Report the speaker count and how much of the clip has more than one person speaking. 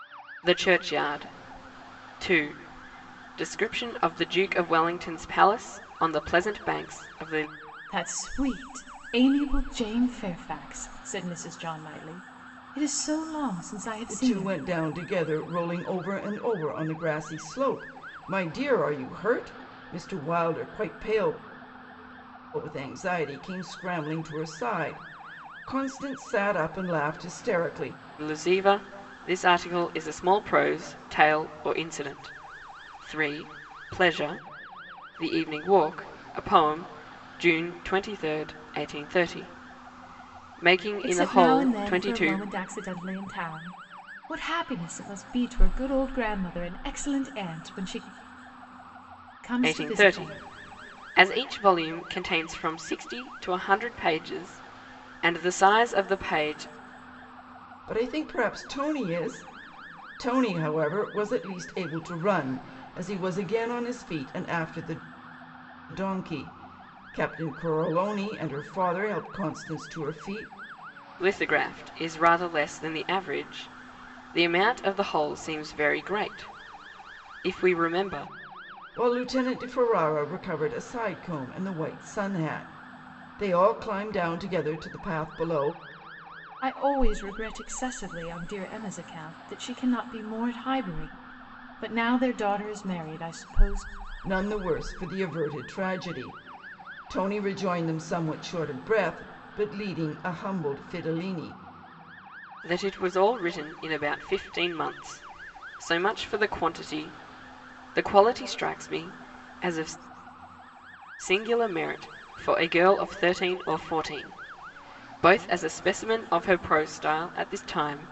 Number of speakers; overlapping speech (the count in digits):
3, about 2%